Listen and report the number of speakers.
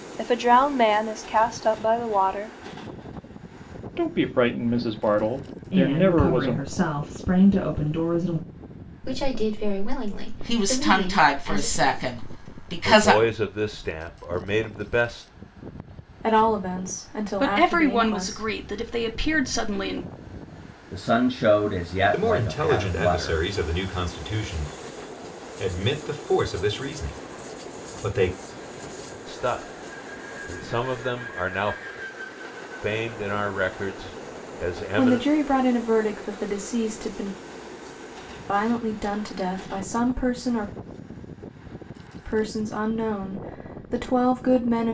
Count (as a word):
ten